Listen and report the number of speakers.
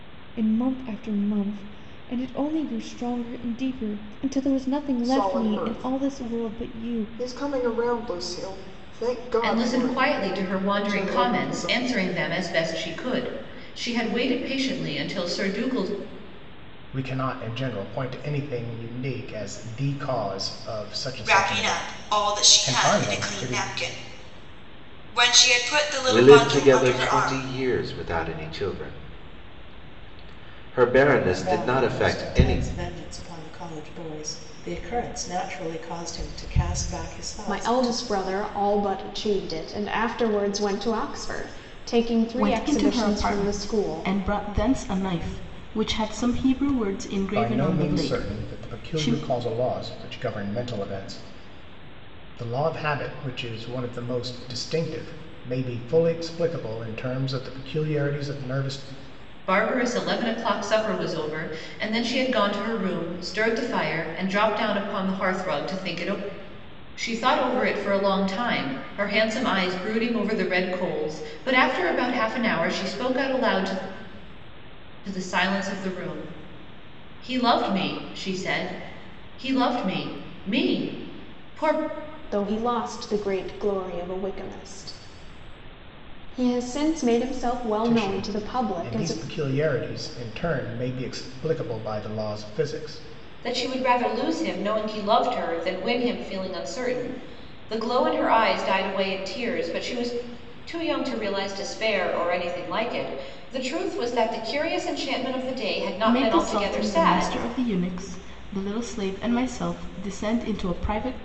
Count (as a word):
nine